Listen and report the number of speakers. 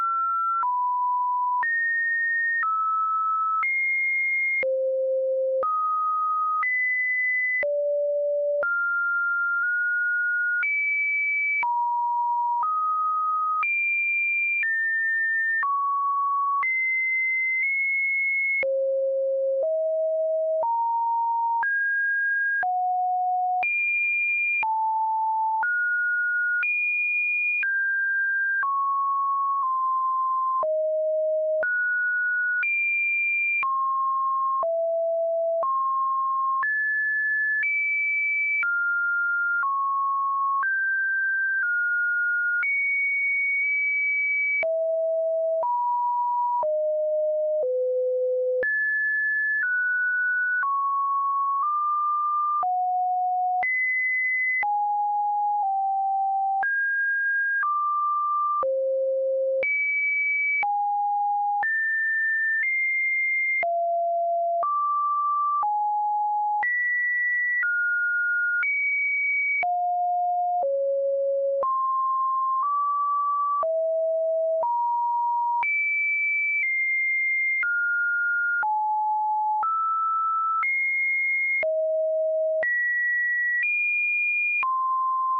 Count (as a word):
zero